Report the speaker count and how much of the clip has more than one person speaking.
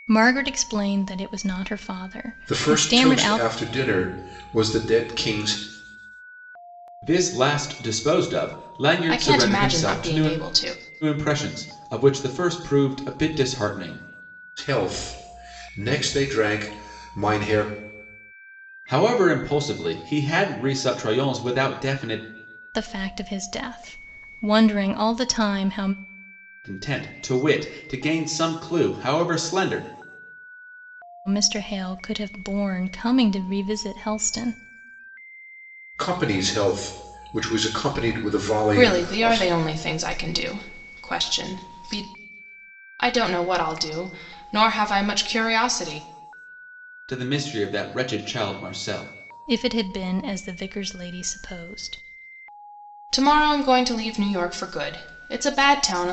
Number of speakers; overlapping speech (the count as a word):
four, about 5%